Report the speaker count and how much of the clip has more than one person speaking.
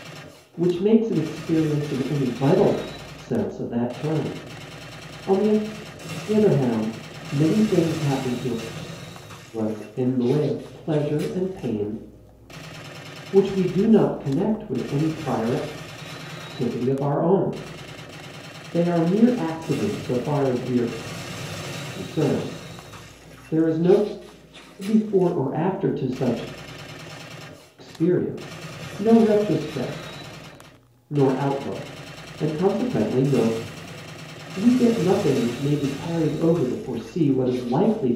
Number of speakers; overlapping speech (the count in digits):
1, no overlap